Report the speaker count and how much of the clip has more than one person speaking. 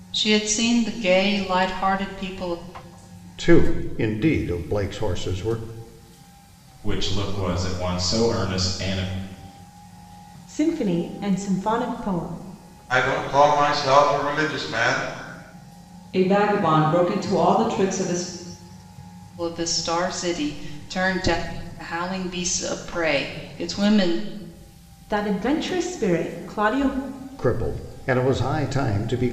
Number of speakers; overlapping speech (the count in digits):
6, no overlap